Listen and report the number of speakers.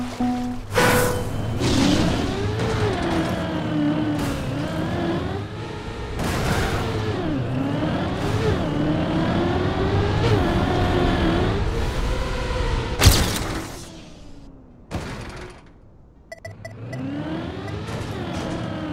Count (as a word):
zero